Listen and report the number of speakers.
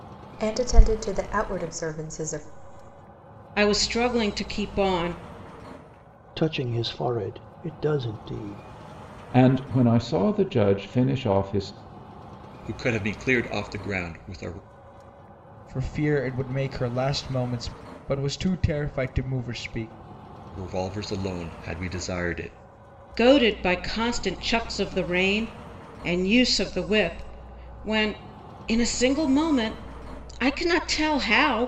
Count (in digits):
6